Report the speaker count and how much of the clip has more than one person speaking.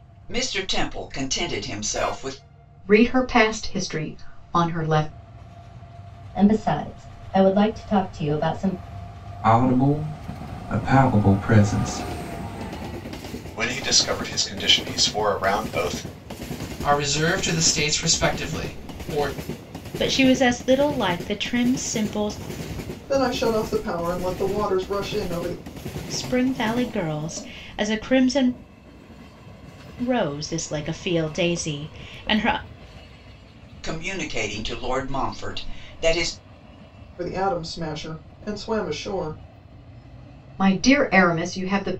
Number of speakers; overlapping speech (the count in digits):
8, no overlap